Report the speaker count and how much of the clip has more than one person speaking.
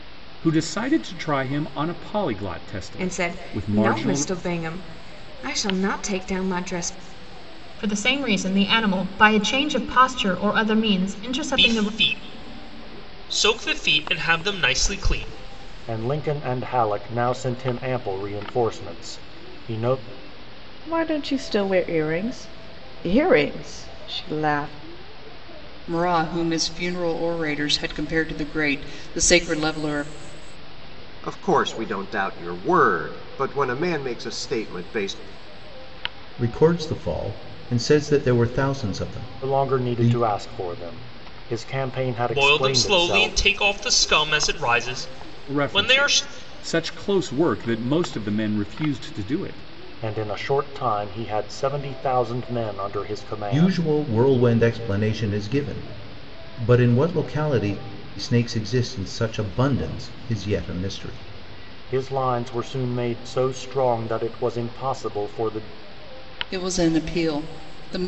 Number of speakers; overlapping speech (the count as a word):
nine, about 7%